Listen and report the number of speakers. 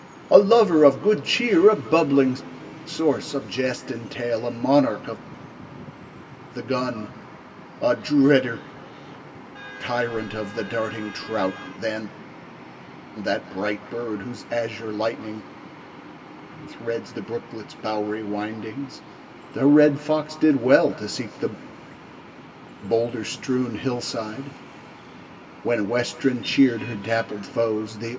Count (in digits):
1